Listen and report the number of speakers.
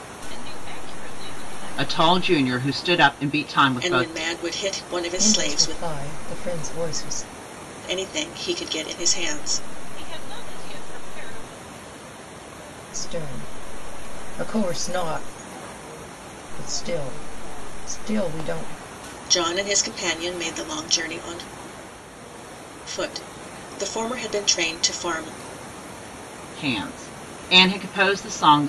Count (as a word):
four